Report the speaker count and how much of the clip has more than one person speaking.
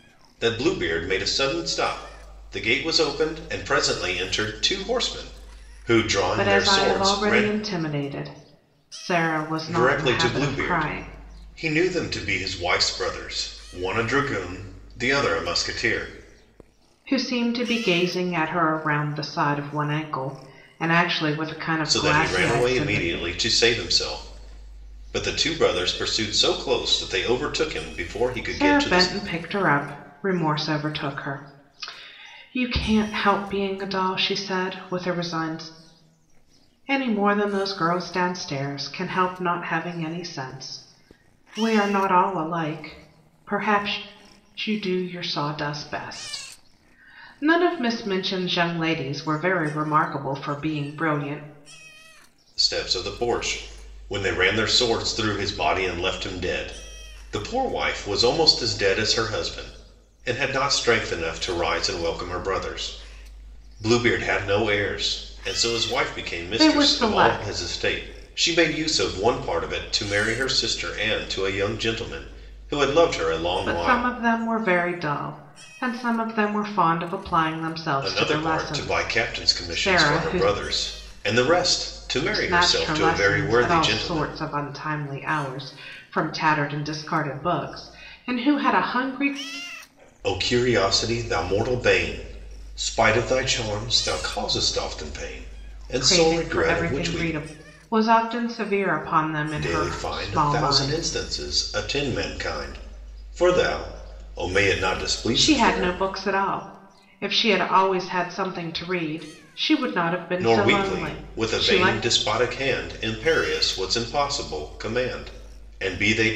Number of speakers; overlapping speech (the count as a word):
two, about 14%